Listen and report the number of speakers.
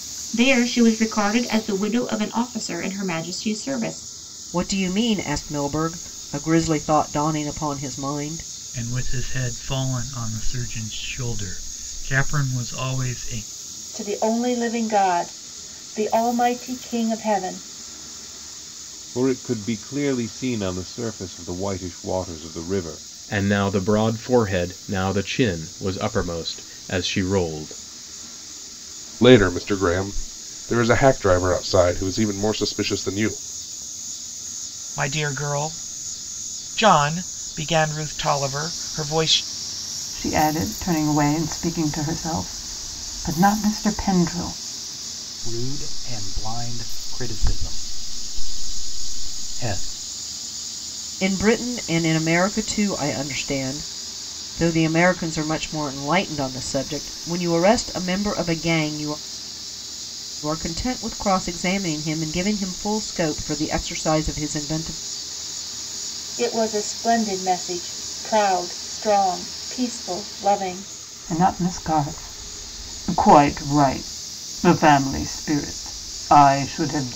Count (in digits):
10